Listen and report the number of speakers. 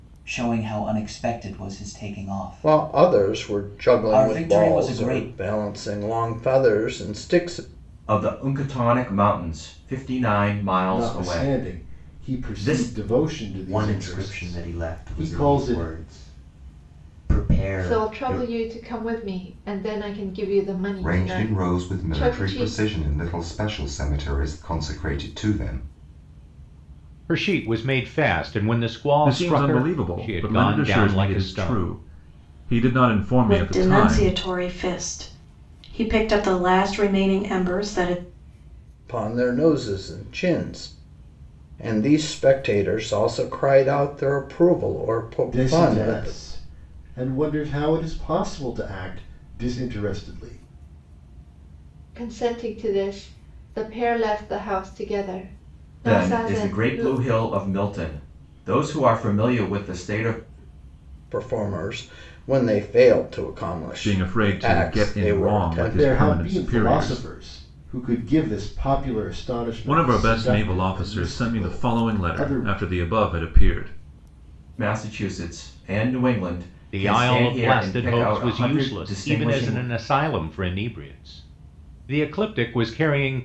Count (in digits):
10